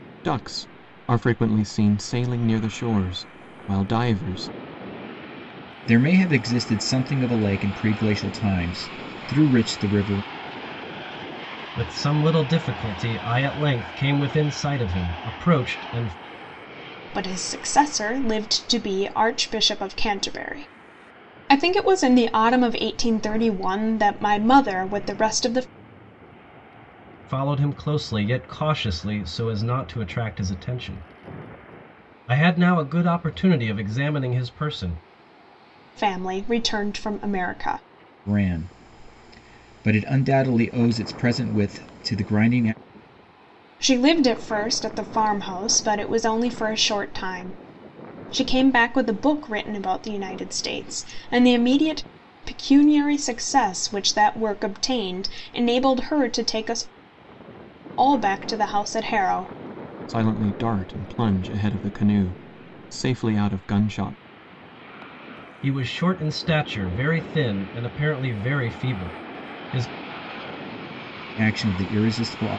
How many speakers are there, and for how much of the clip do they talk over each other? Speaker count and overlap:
four, no overlap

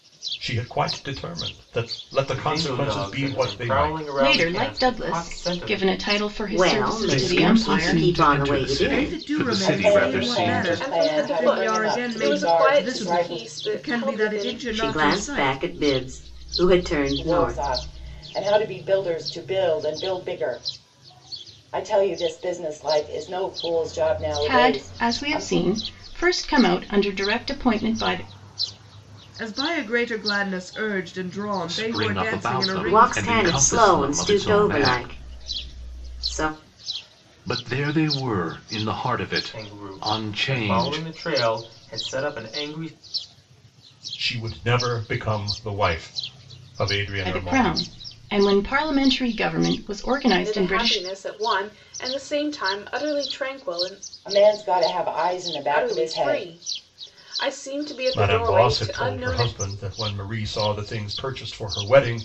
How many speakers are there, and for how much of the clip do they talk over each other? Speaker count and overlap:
eight, about 38%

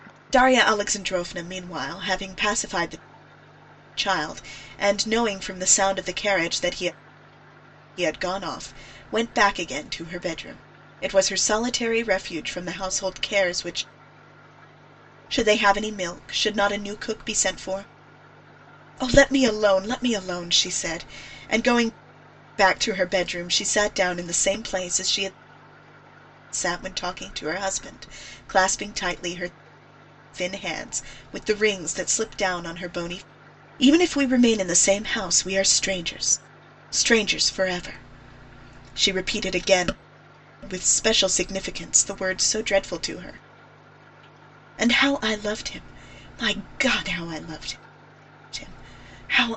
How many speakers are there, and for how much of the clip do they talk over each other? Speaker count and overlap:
one, no overlap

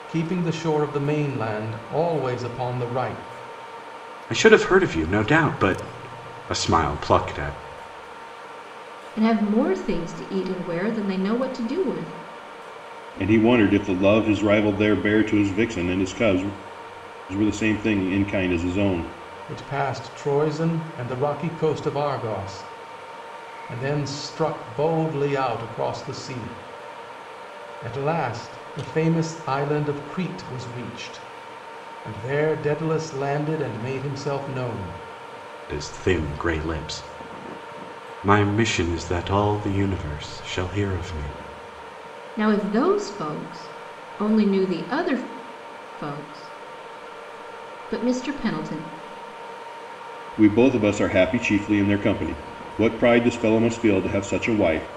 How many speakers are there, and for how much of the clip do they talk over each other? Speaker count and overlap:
four, no overlap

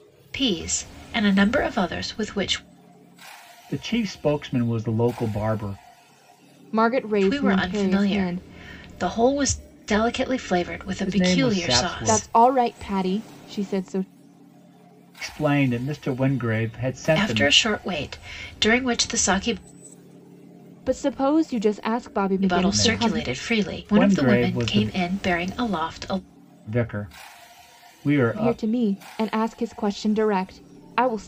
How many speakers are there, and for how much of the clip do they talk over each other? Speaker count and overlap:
three, about 22%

